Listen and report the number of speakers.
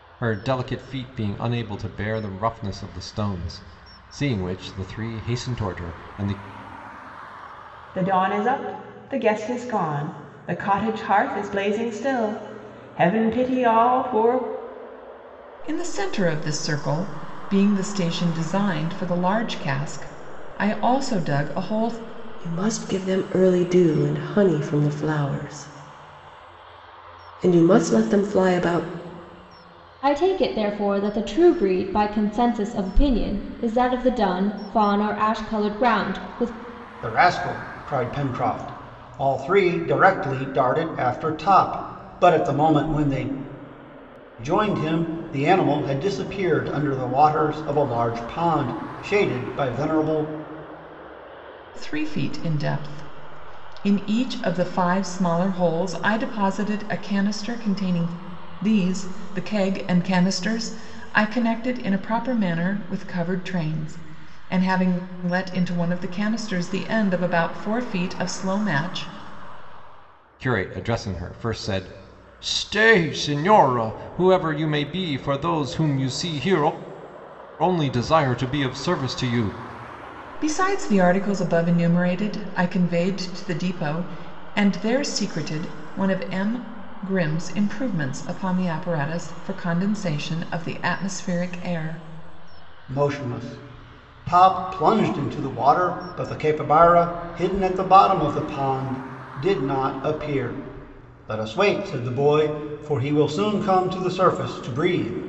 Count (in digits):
6